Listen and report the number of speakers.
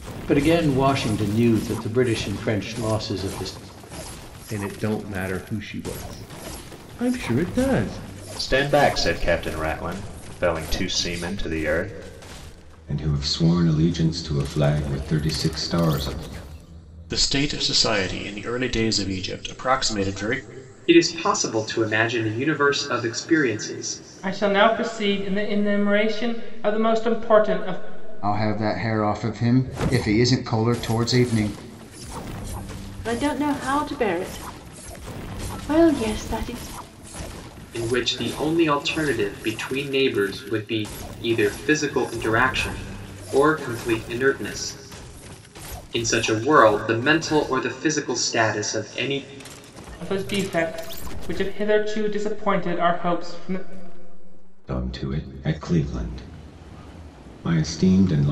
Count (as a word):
nine